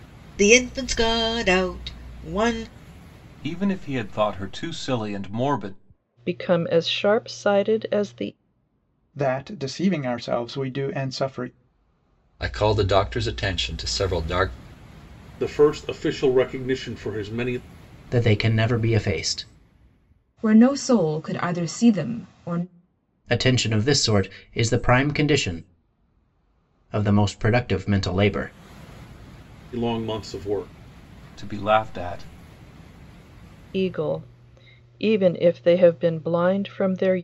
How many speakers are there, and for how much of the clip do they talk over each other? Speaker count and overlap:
8, no overlap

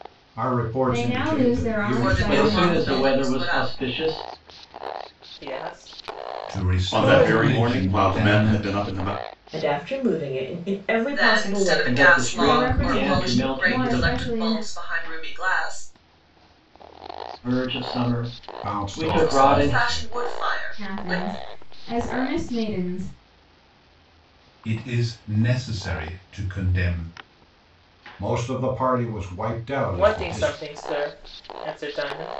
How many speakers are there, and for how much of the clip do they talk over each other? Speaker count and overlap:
8, about 35%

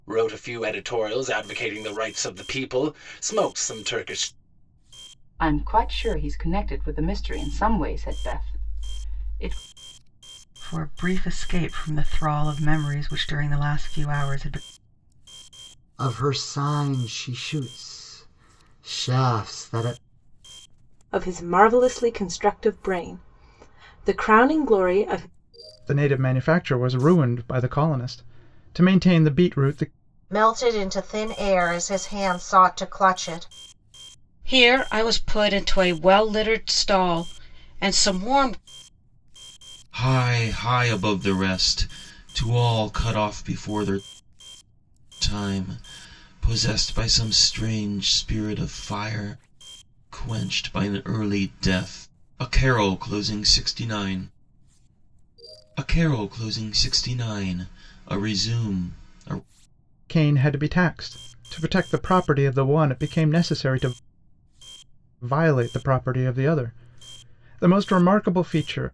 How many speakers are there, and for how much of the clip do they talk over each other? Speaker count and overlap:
9, no overlap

